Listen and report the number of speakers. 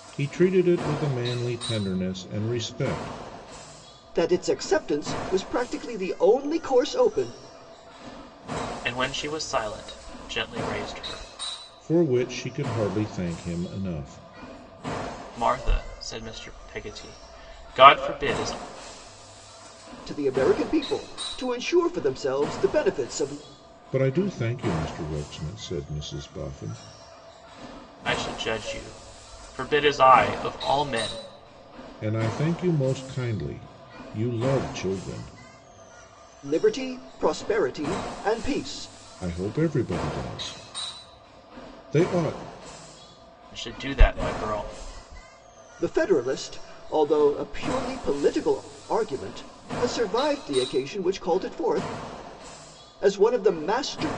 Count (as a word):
three